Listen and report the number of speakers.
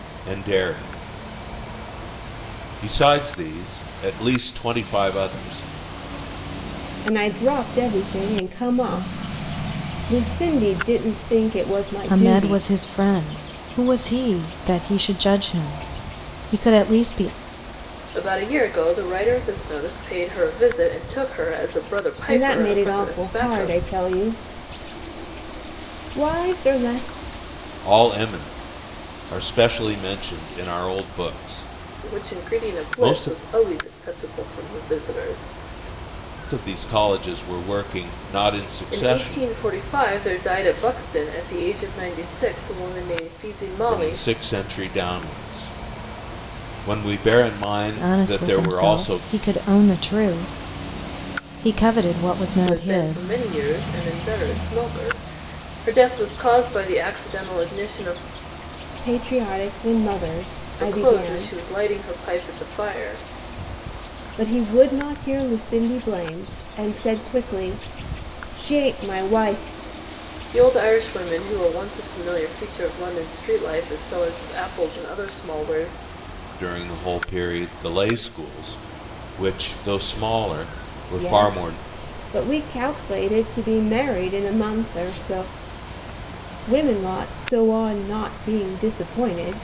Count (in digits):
4